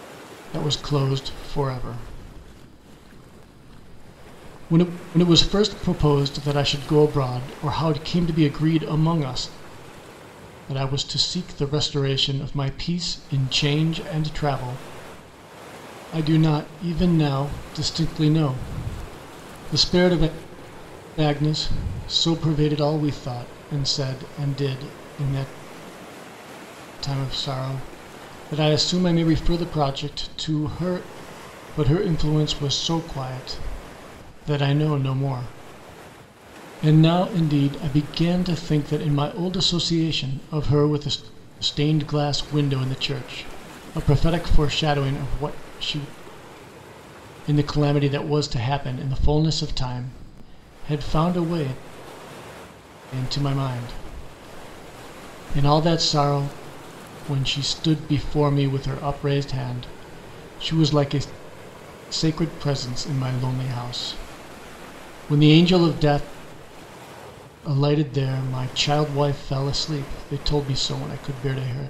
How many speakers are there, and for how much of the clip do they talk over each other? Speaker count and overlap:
one, no overlap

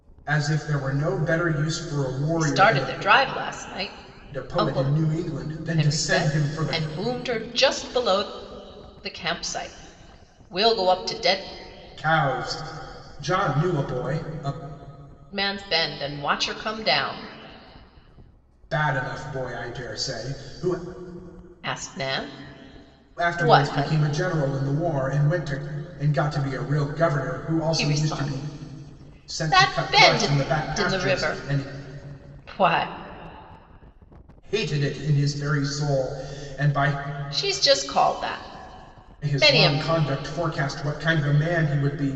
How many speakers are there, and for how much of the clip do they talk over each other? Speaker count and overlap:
two, about 16%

